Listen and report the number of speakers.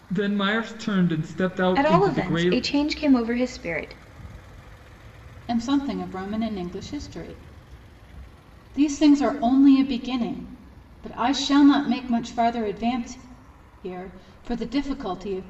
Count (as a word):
three